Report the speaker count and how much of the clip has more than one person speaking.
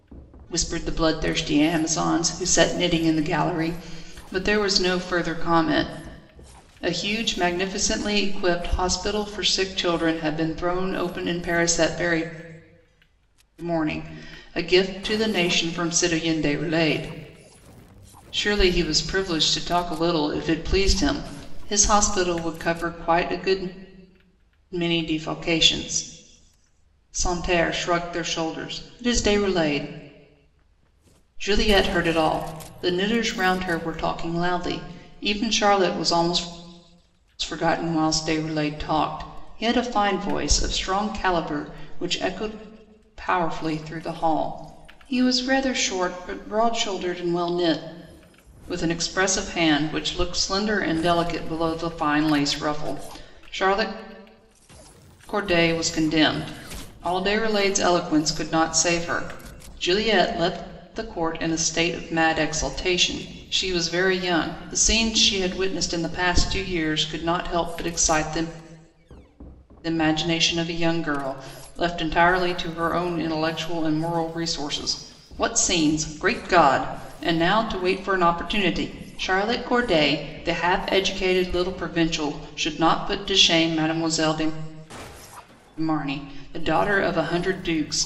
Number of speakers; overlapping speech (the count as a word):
one, no overlap